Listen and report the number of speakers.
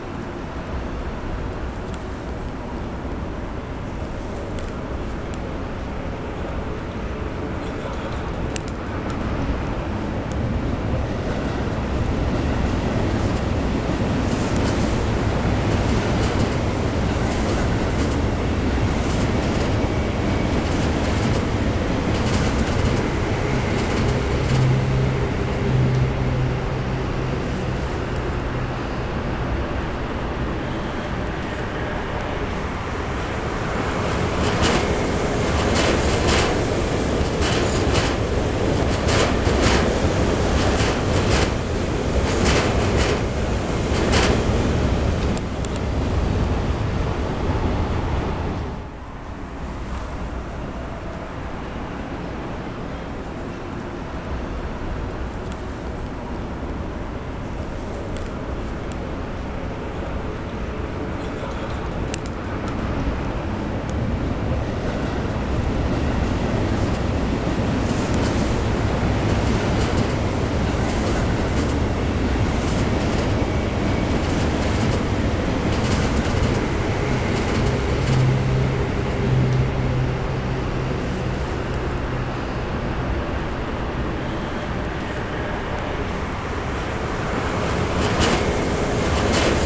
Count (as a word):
zero